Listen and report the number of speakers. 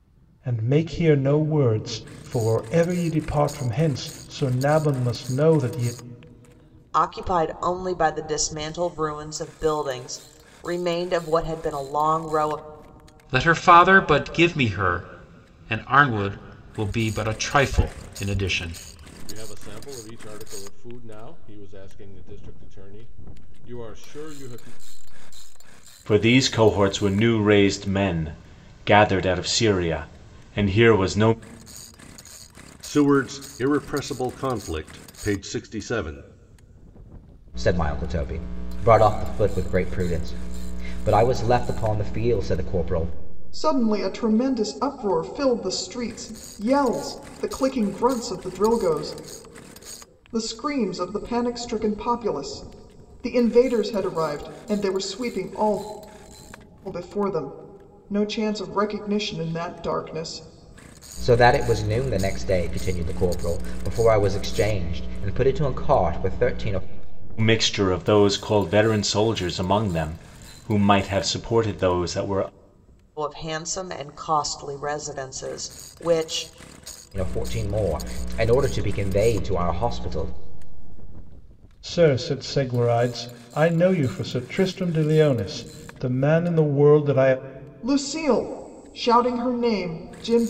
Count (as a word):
eight